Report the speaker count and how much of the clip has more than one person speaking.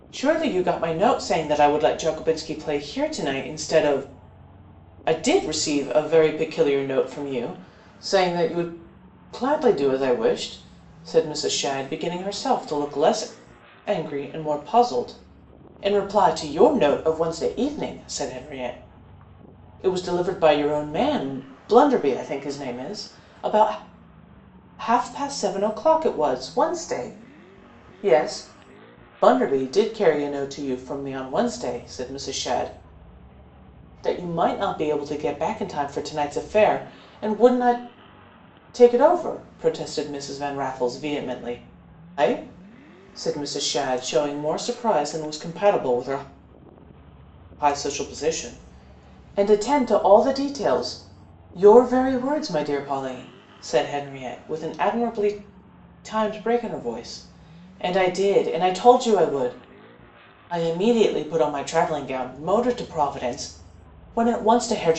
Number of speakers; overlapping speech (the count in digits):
1, no overlap